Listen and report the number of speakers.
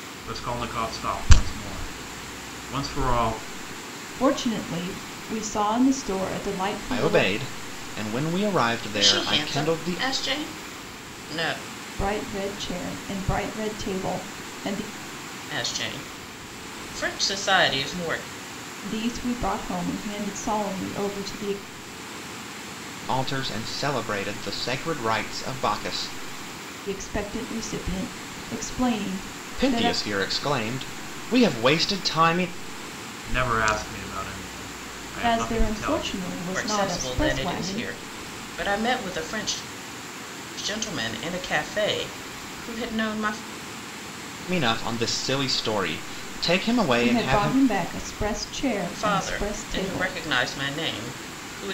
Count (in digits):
4